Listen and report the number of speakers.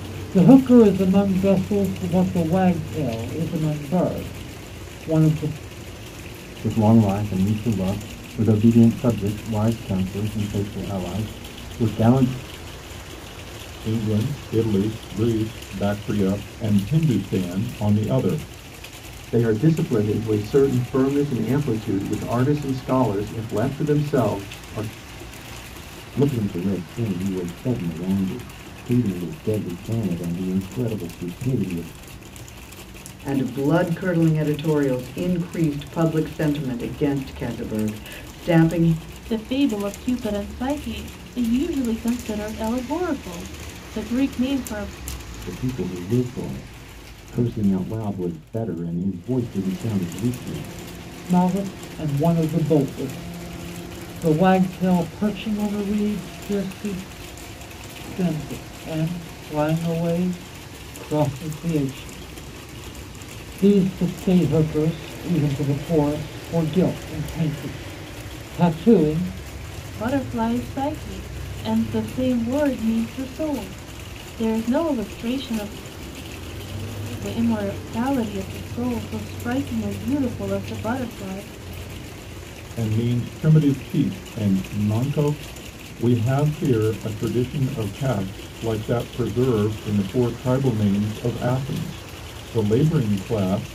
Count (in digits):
7